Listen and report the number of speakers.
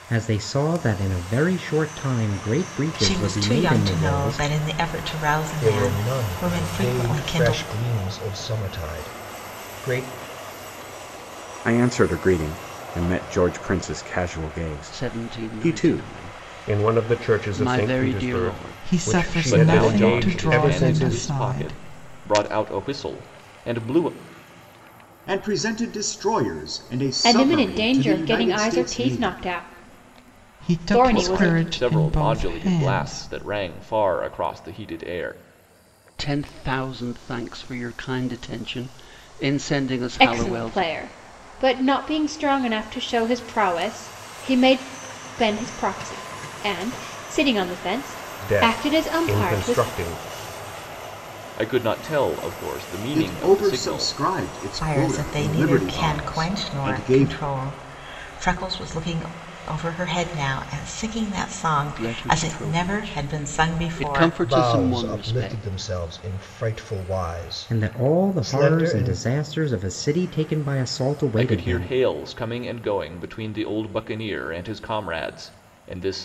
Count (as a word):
ten